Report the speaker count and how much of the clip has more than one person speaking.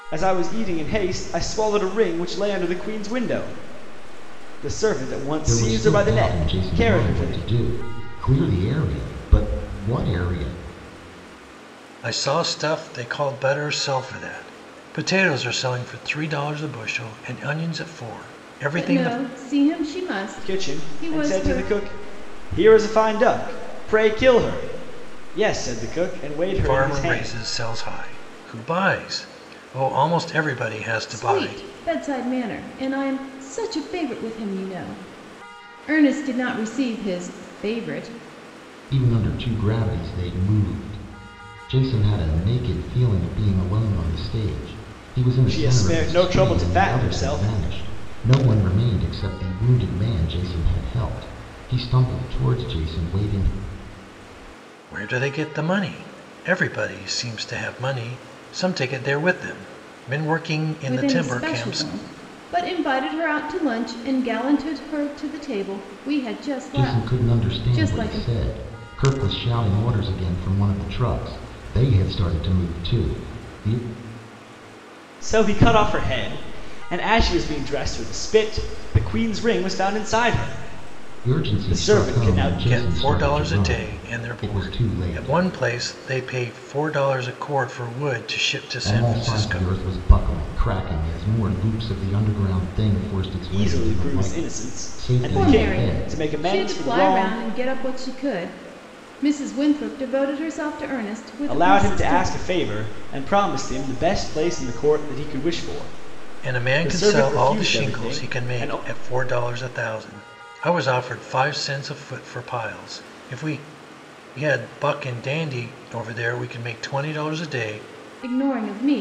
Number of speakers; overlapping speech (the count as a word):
four, about 19%